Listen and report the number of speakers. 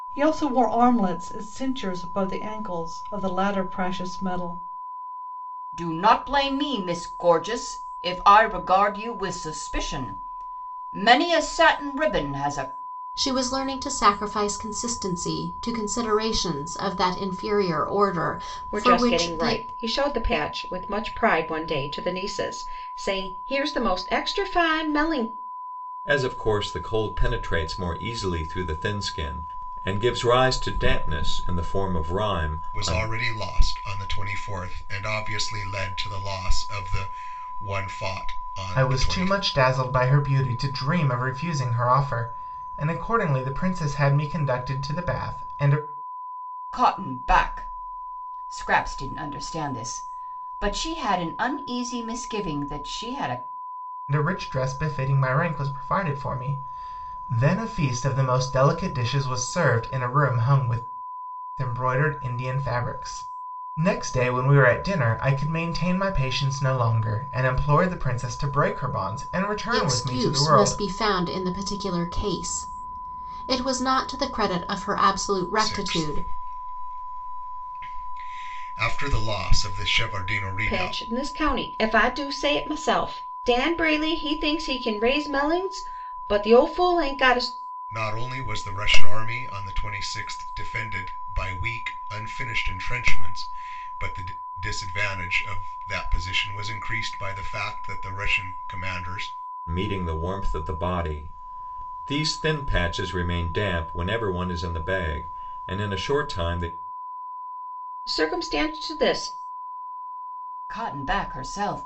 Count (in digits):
7